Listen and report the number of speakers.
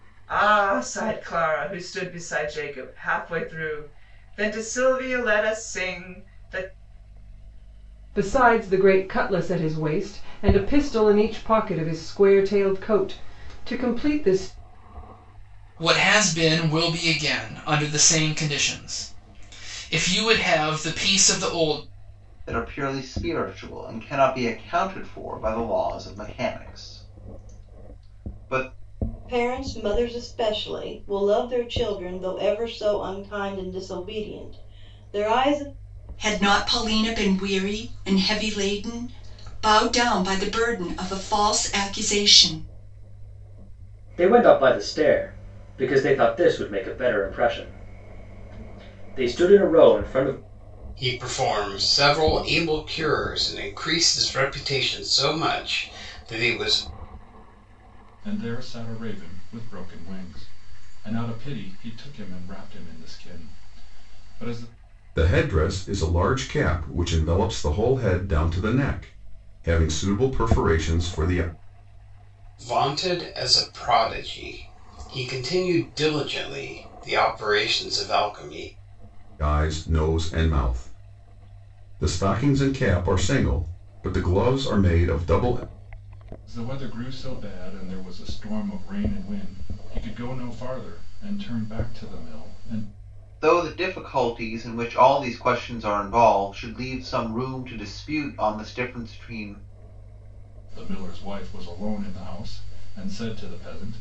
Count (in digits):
10